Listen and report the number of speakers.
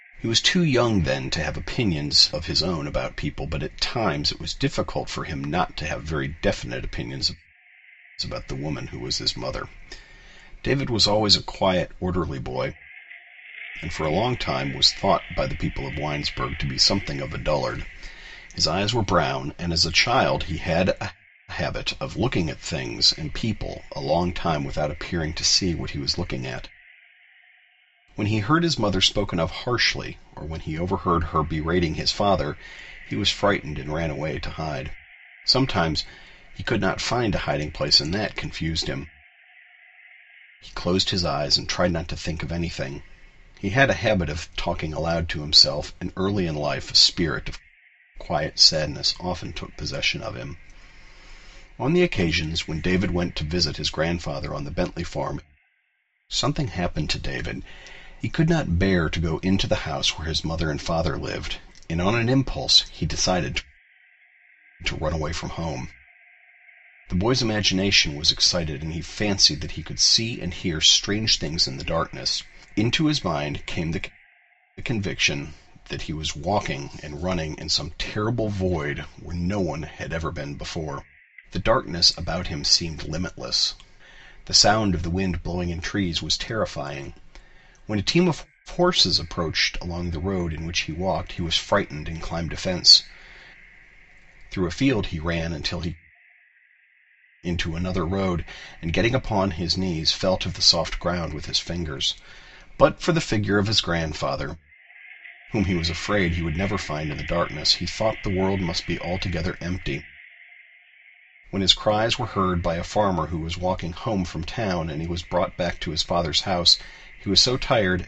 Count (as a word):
one